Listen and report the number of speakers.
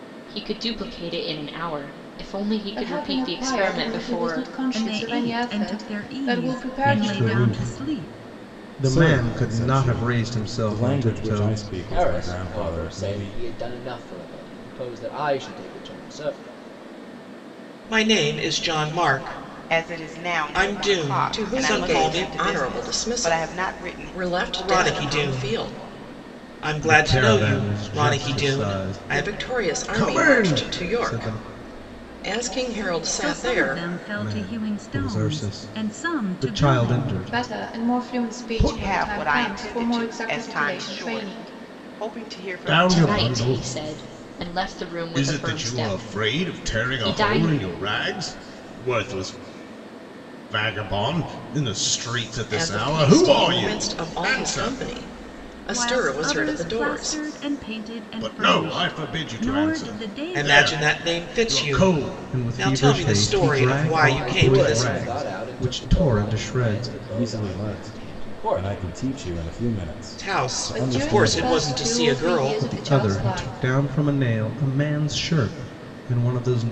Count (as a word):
nine